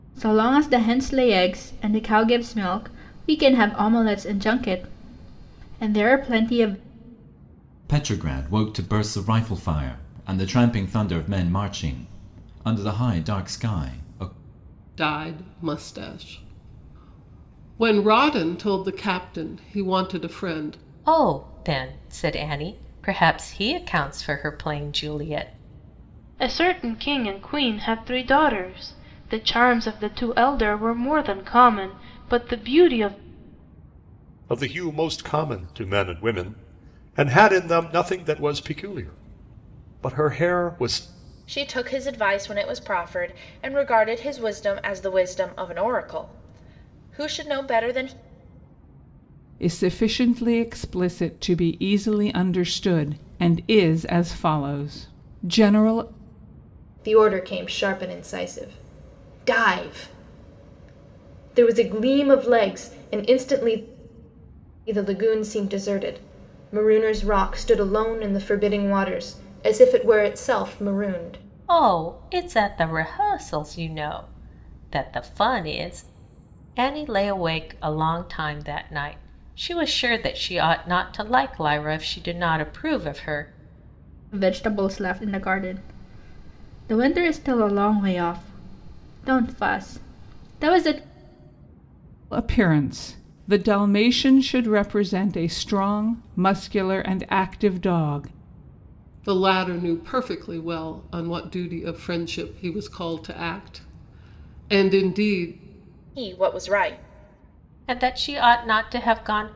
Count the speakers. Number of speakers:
9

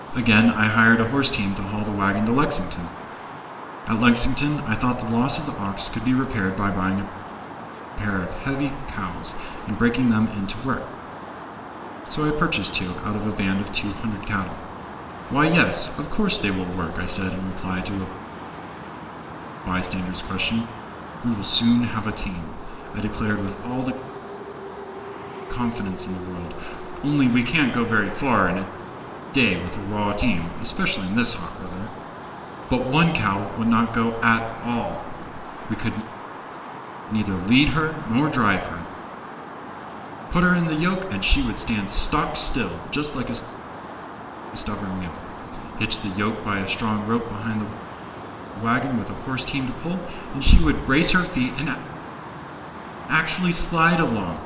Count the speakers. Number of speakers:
1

